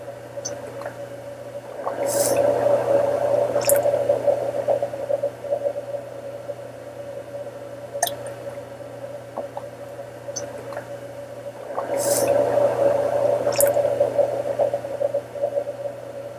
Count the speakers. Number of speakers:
0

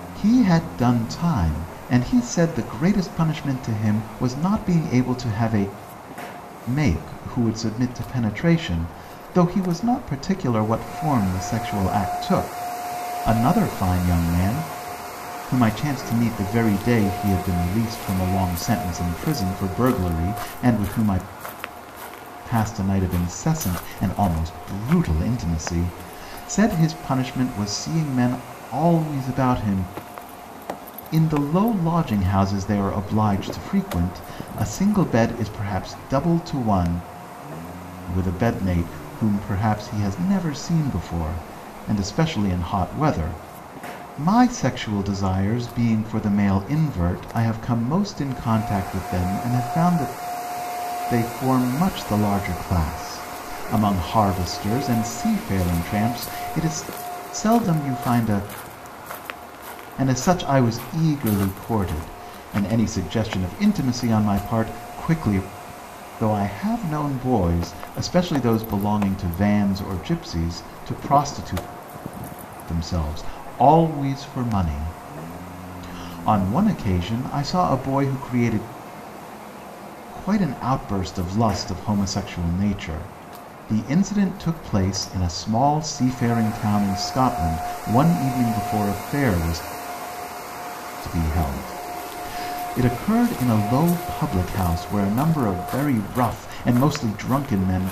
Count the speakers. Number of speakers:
1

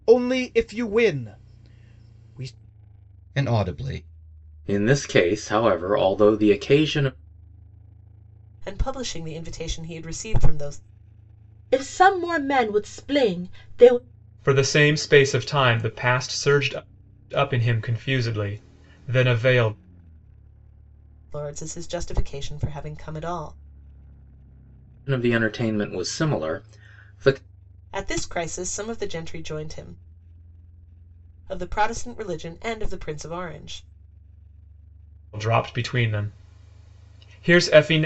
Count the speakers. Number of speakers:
6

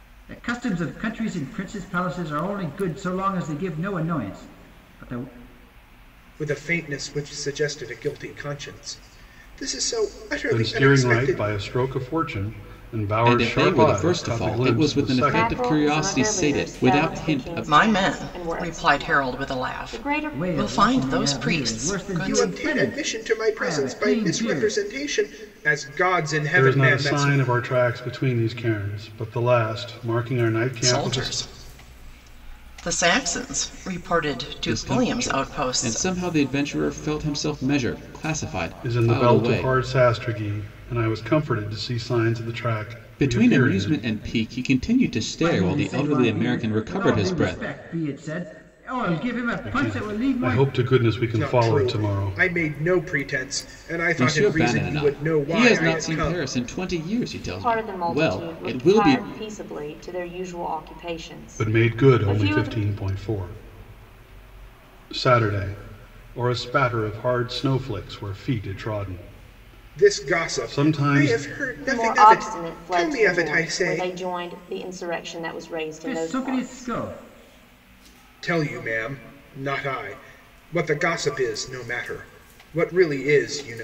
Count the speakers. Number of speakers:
6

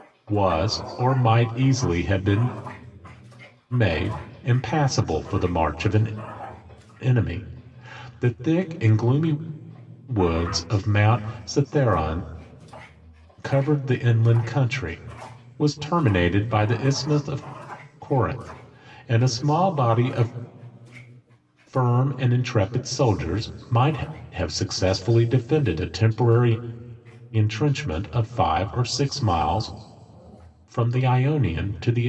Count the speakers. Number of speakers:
1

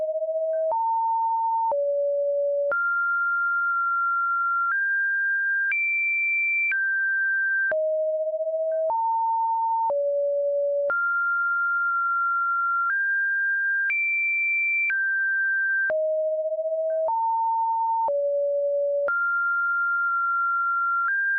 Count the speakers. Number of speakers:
0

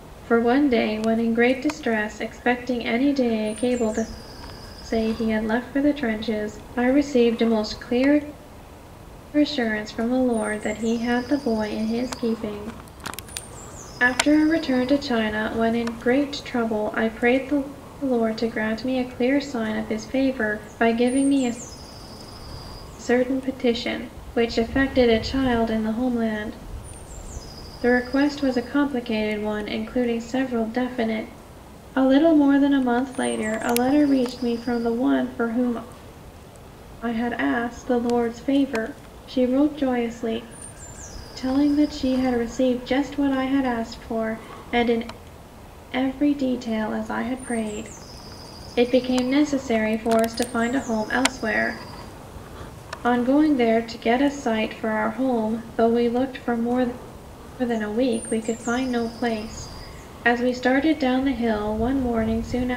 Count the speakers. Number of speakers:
1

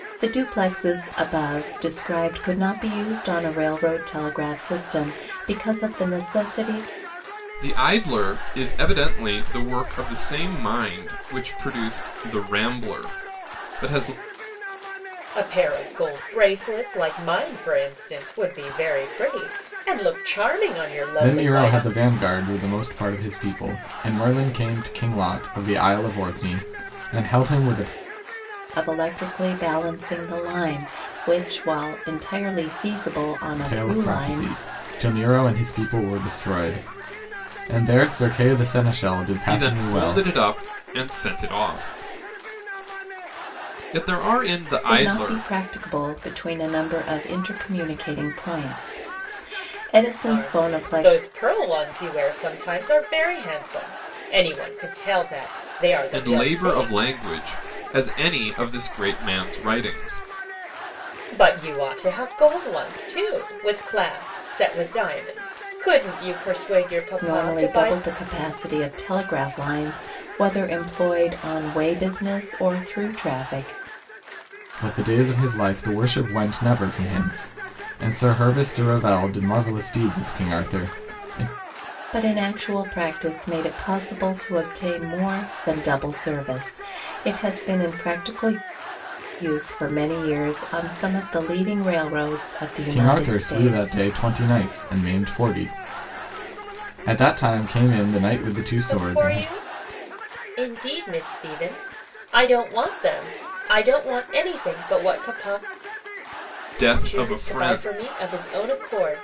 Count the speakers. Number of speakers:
4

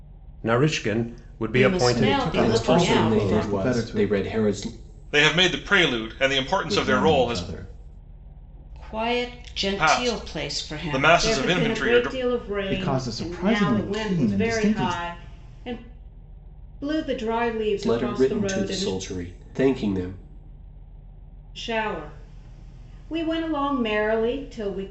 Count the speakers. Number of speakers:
5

